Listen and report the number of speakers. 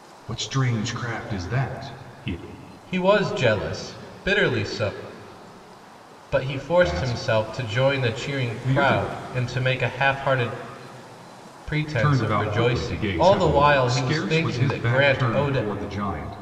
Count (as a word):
two